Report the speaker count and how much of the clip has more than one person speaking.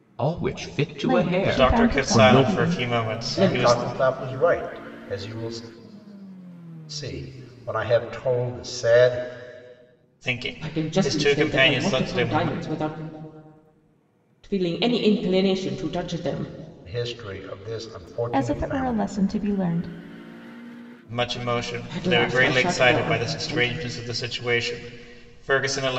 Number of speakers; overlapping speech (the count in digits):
5, about 28%